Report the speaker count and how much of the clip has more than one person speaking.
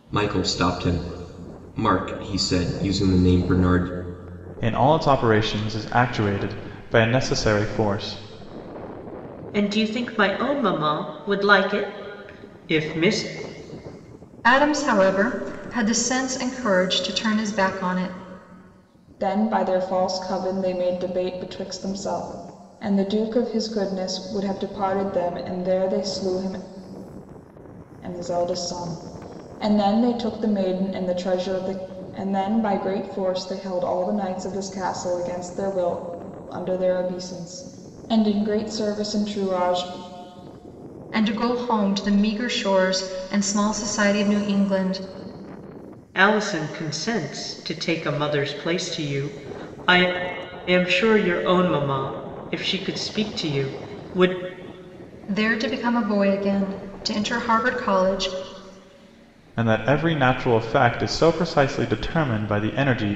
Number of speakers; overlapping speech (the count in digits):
5, no overlap